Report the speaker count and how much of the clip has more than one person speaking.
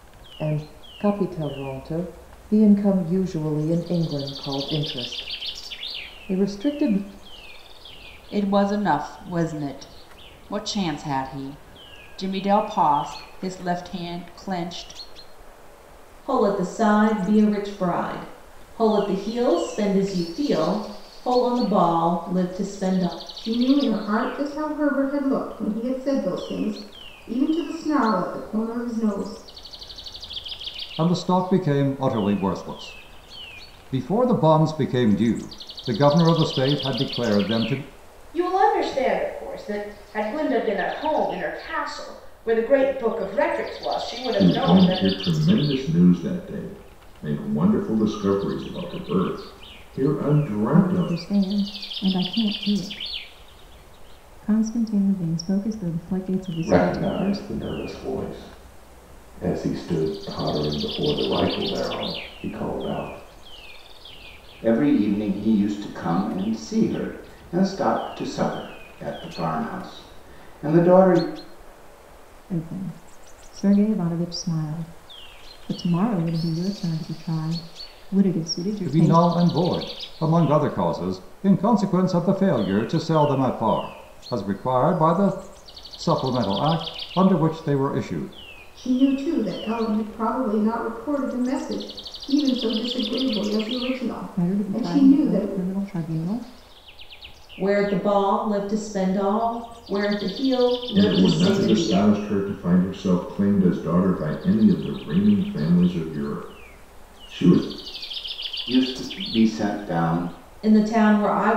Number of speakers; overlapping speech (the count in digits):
10, about 5%